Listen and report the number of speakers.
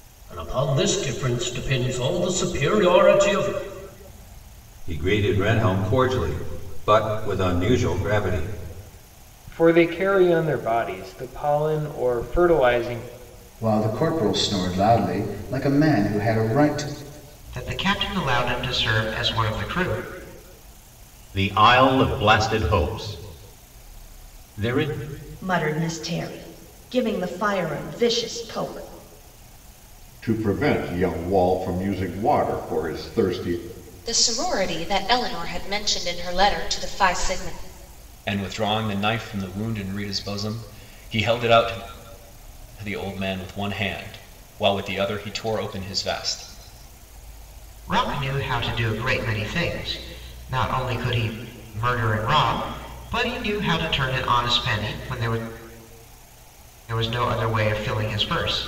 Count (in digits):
10